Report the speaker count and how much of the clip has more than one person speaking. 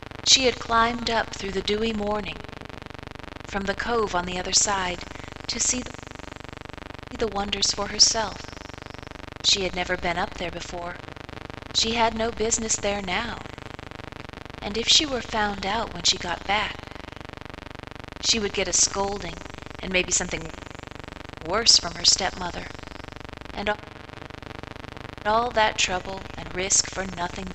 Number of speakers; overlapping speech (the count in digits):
1, no overlap